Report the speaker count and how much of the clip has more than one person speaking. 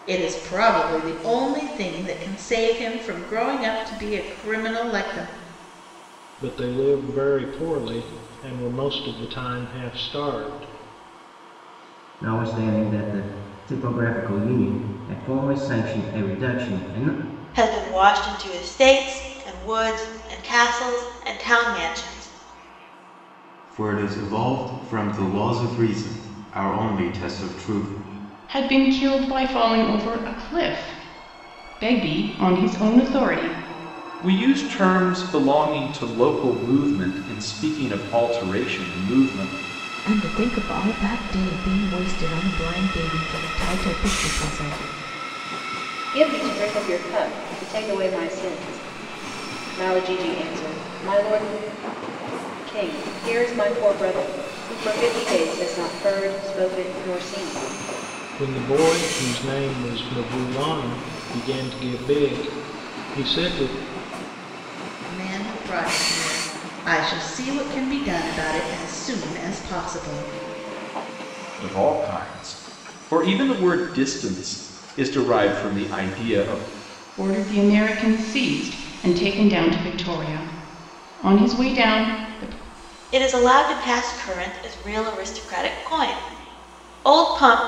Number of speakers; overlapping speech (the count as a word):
nine, no overlap